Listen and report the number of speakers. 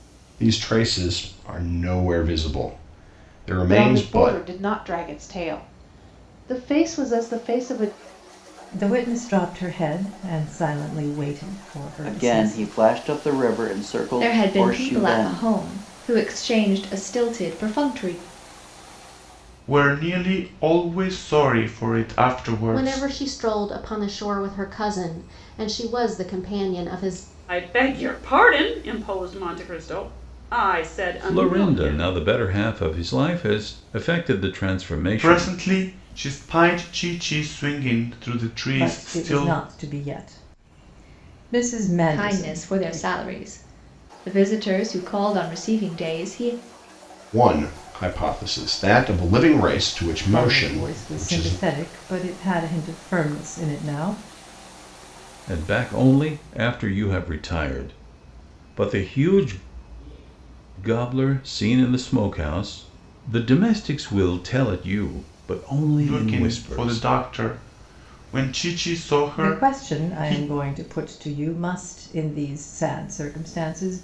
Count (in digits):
9